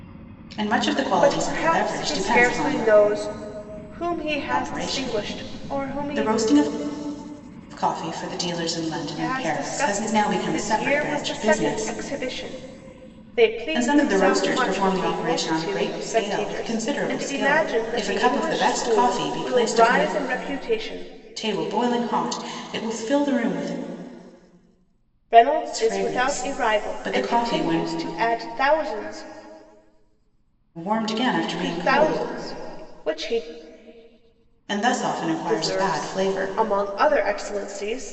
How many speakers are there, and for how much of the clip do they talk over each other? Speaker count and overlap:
2, about 44%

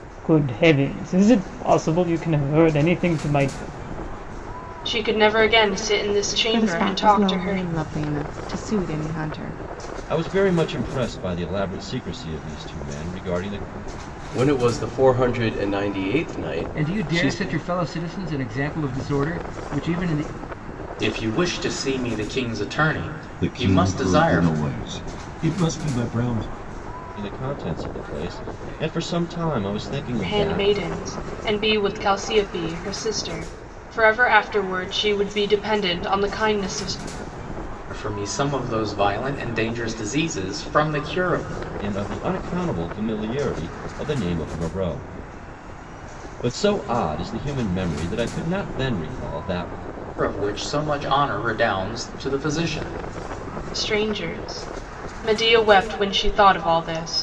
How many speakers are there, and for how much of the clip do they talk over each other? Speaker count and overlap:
8, about 6%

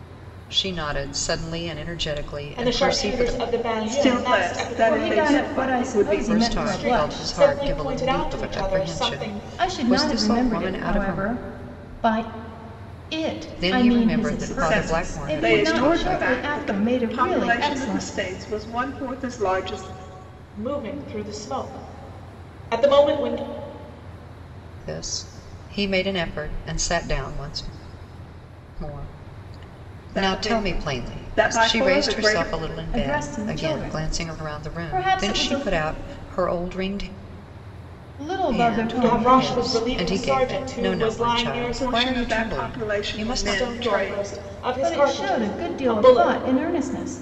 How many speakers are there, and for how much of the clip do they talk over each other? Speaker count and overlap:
4, about 54%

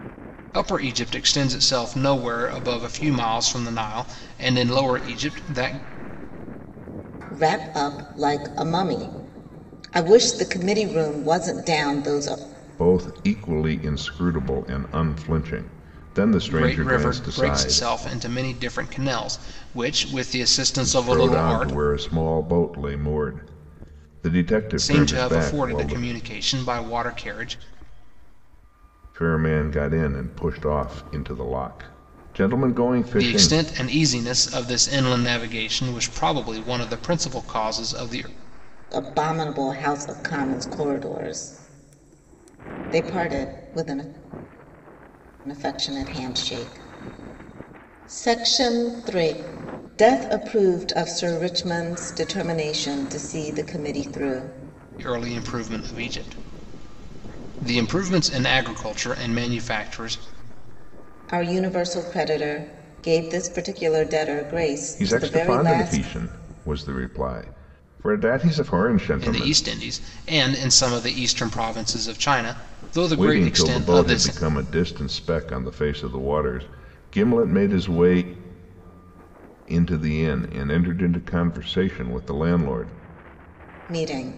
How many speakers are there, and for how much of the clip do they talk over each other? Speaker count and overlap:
3, about 8%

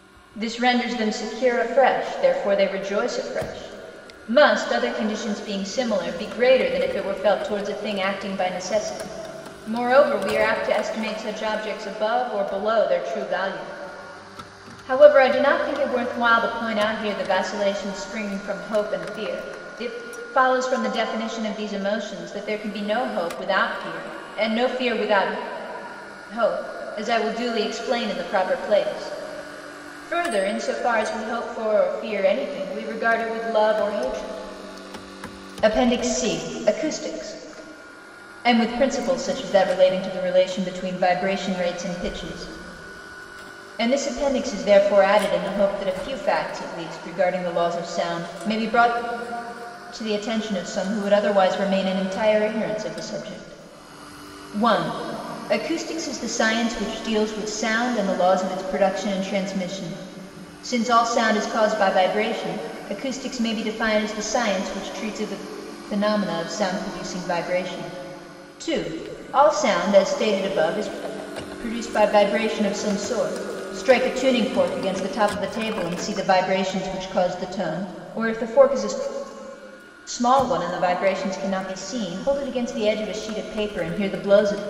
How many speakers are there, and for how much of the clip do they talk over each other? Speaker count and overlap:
1, no overlap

